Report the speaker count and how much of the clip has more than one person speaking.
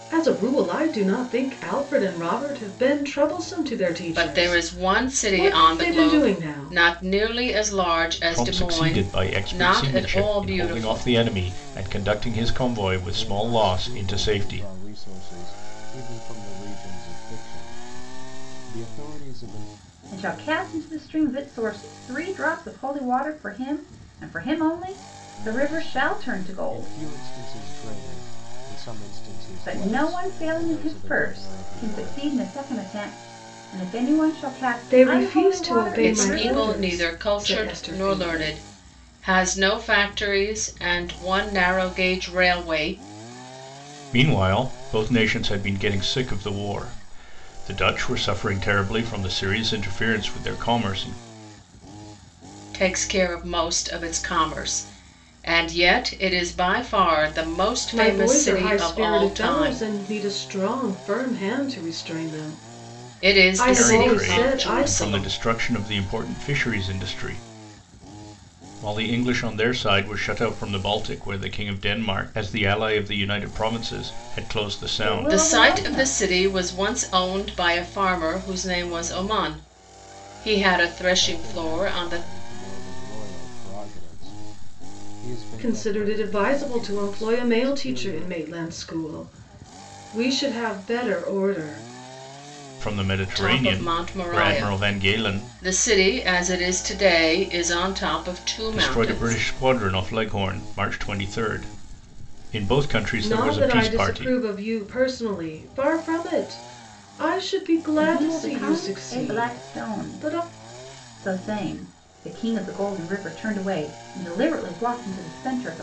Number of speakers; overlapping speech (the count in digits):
5, about 27%